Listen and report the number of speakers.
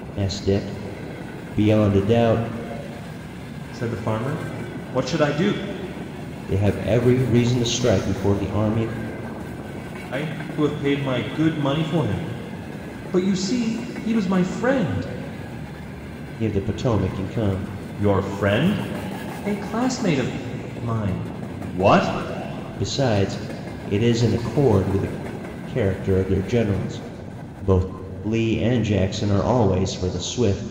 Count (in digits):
2